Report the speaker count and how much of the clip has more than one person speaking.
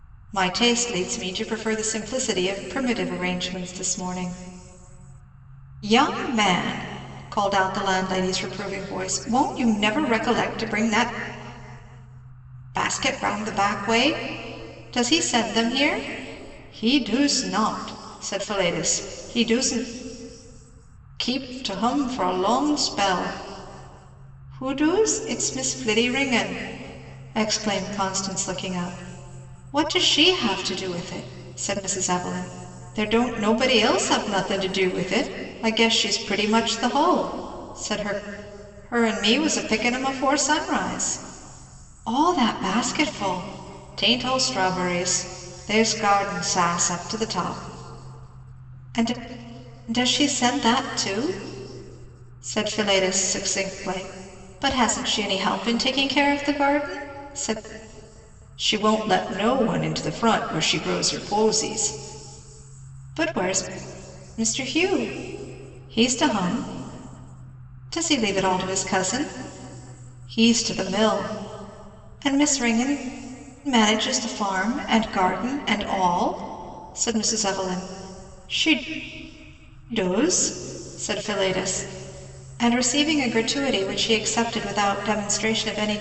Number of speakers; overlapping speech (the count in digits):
1, no overlap